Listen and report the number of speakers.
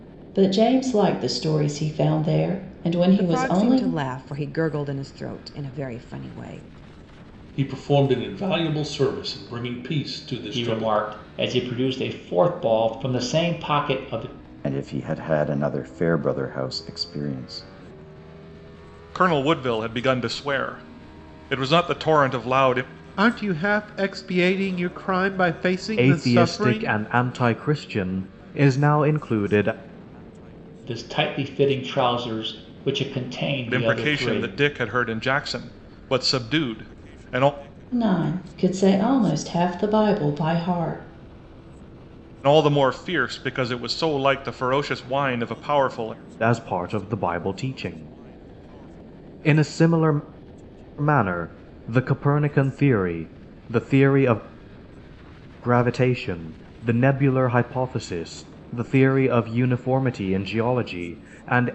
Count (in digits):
8